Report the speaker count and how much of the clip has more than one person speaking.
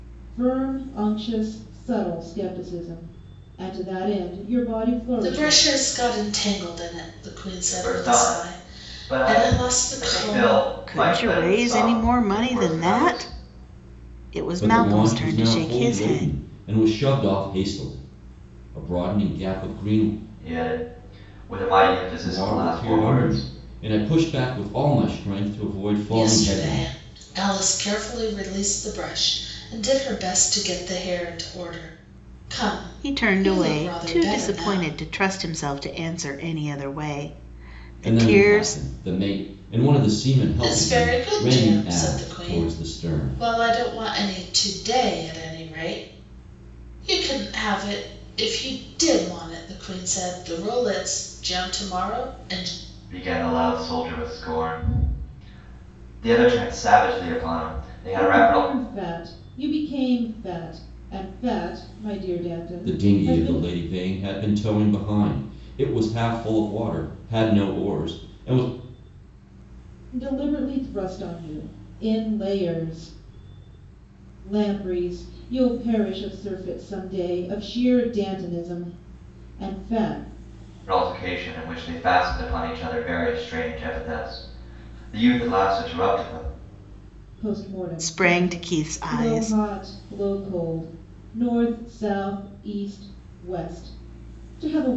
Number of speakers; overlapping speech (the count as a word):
five, about 19%